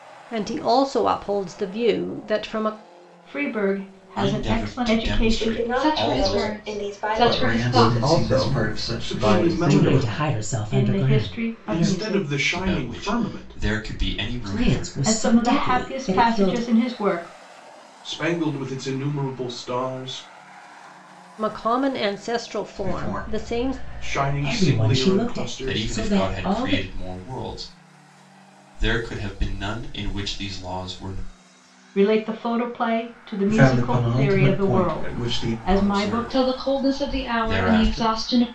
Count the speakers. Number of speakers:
nine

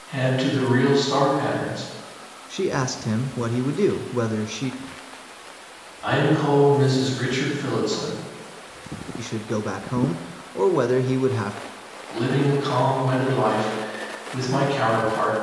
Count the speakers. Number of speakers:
two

